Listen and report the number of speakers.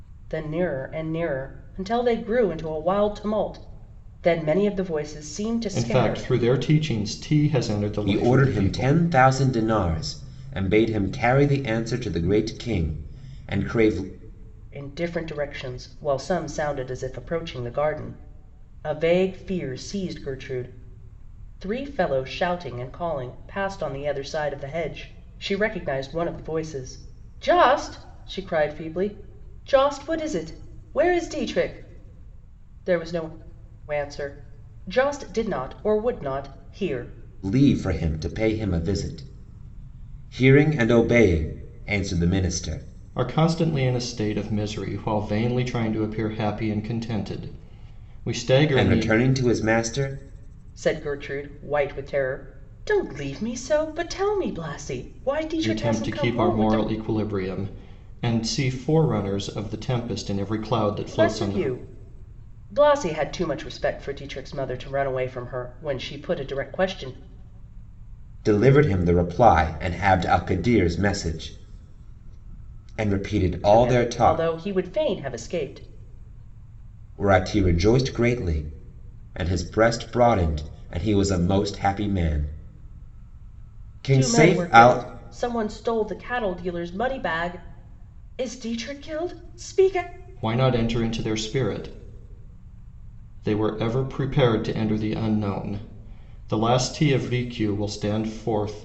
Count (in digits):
3